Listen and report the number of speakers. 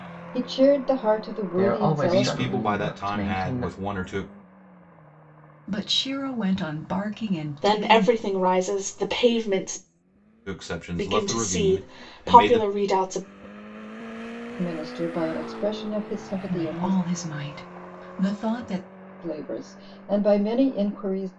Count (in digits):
5